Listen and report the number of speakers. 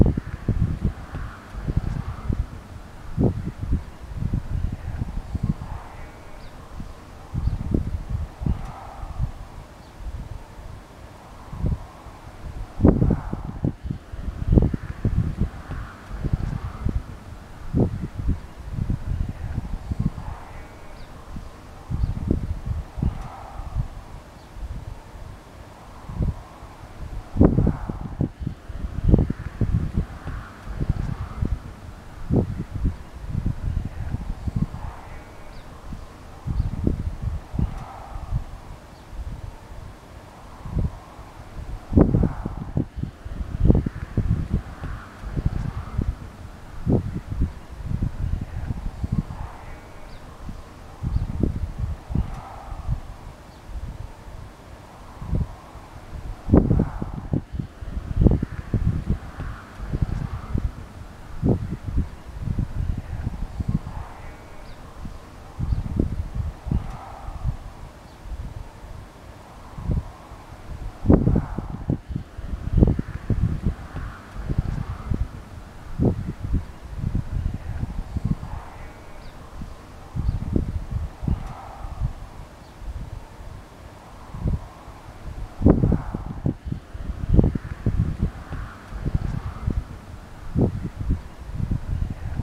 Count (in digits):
0